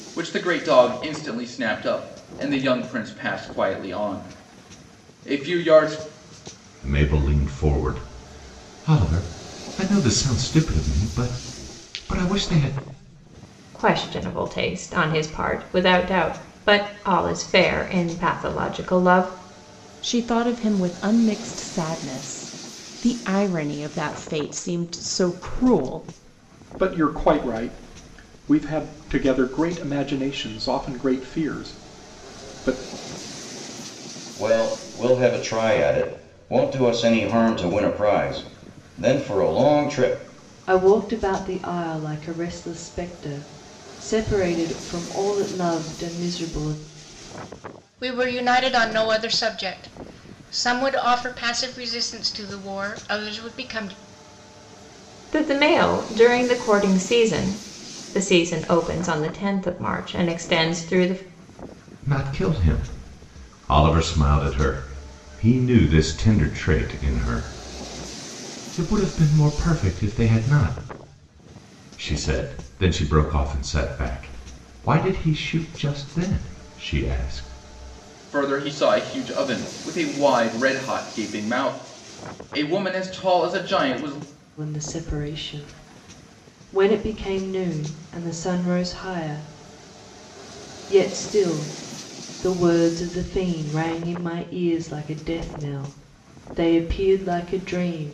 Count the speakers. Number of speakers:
8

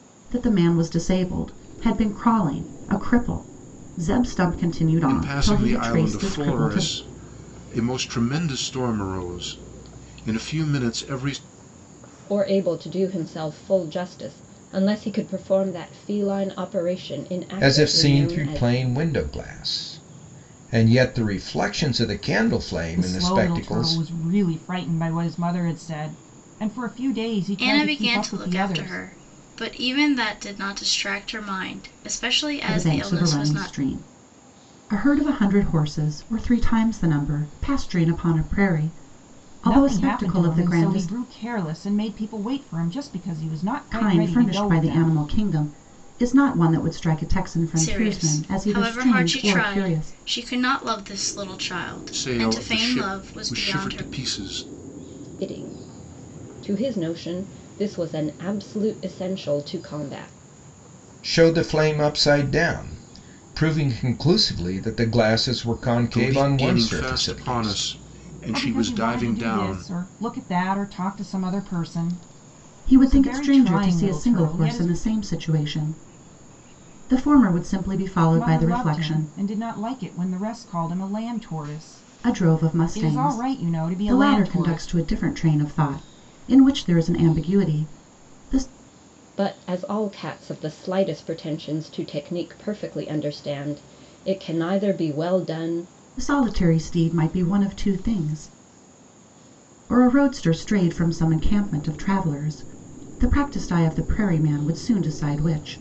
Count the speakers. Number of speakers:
6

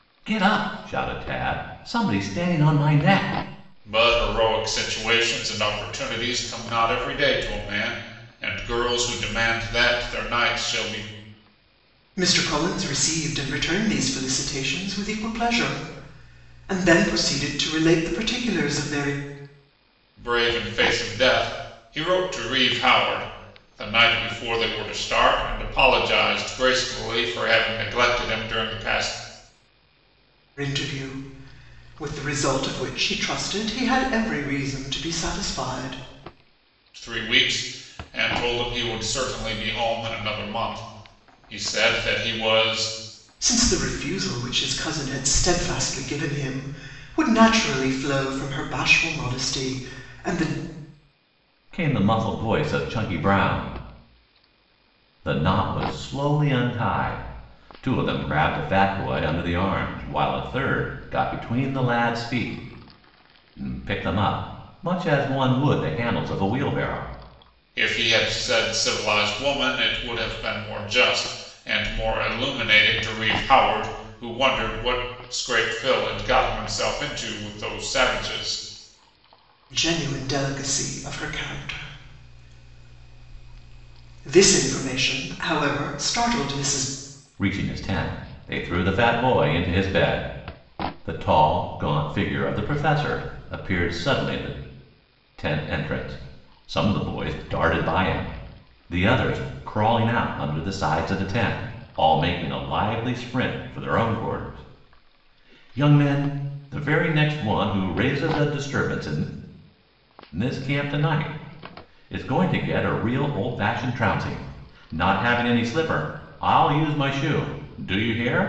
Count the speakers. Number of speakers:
3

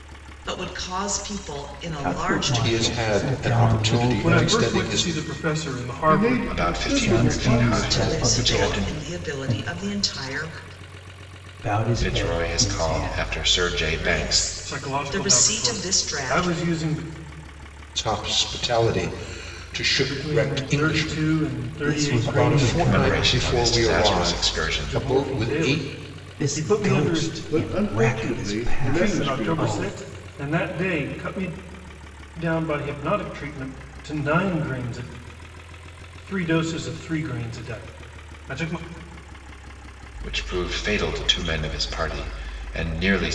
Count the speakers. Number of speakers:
6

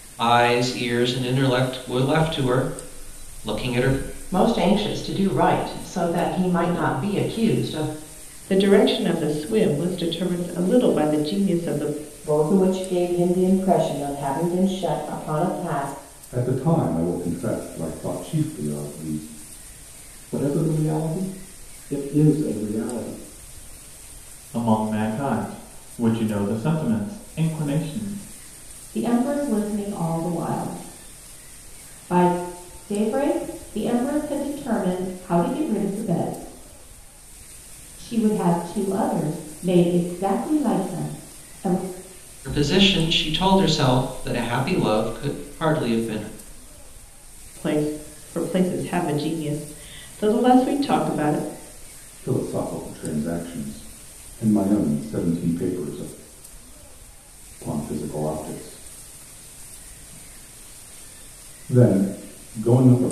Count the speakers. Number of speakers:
8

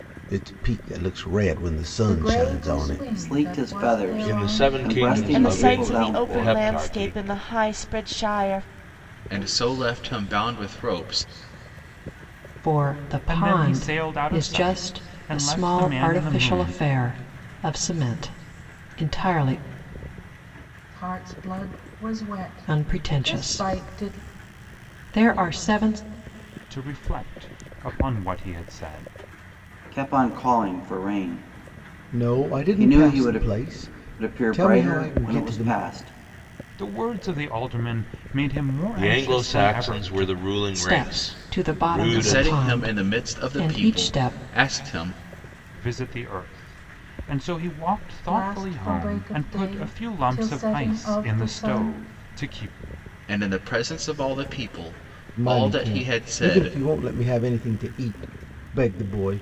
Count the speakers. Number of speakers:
8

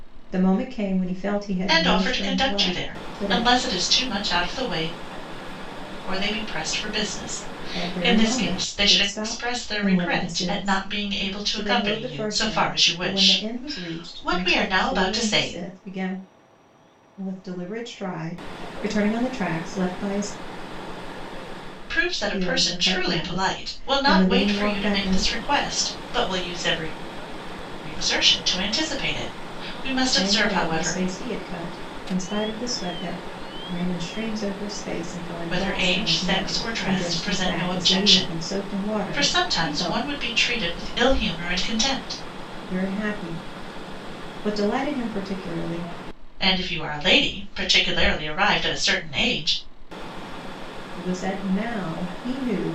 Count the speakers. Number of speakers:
2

